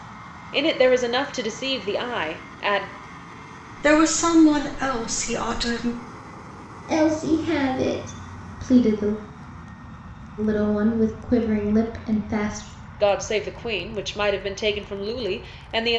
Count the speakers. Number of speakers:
3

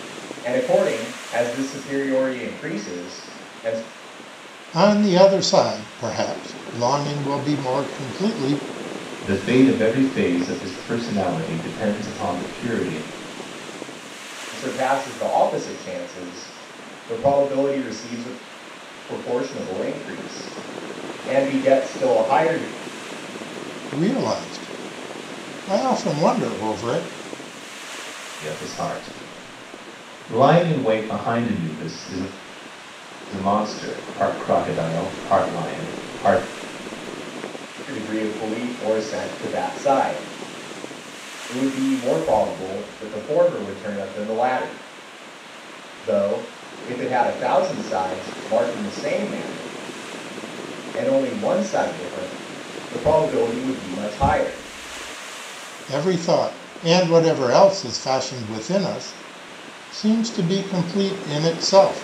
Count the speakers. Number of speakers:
3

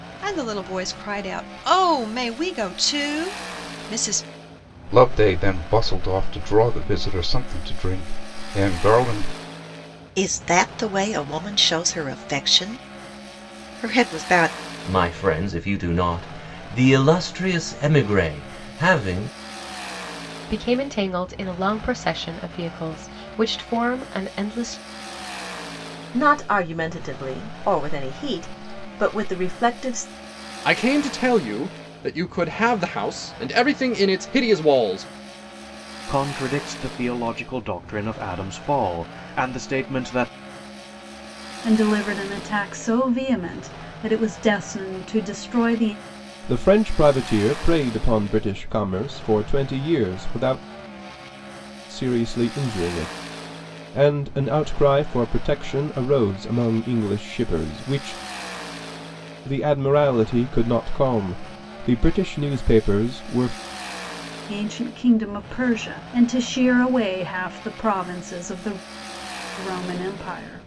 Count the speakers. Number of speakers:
10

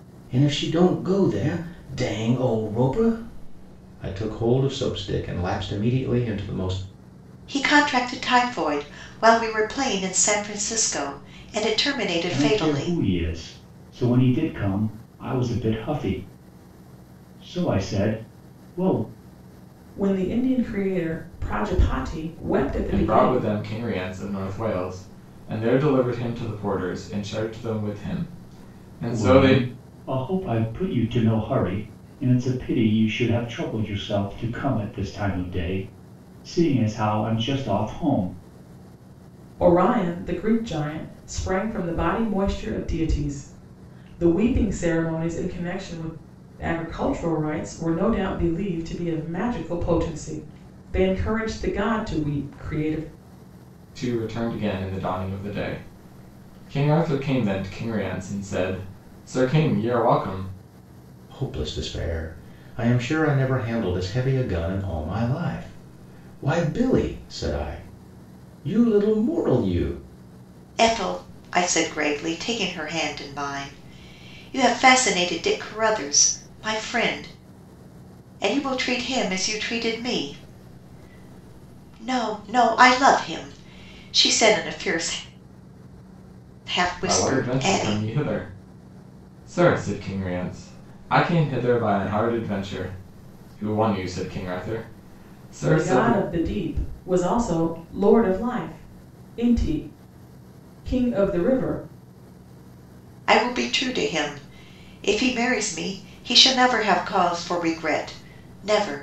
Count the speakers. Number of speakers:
5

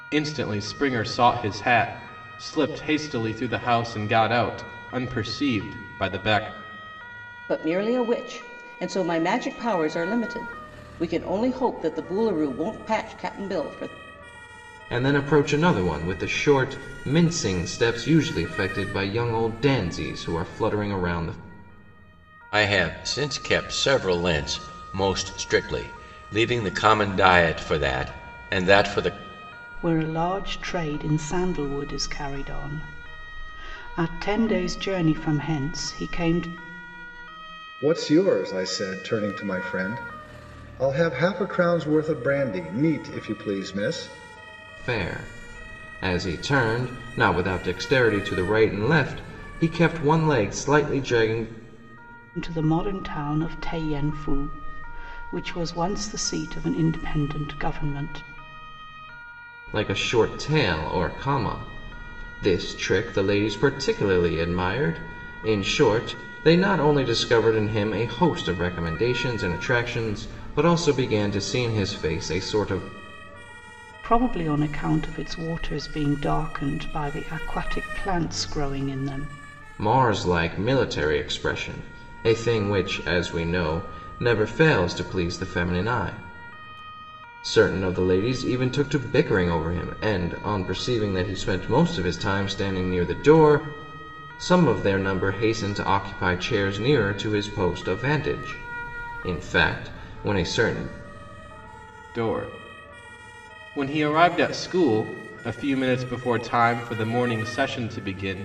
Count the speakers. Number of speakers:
6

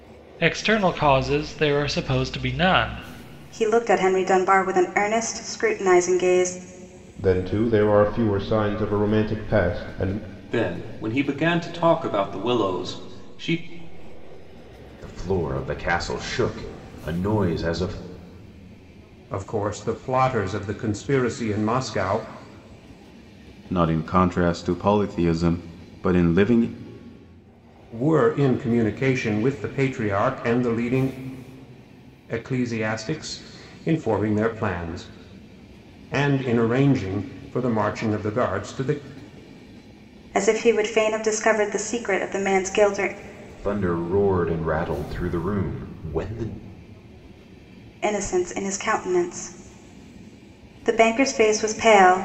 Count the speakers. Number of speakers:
7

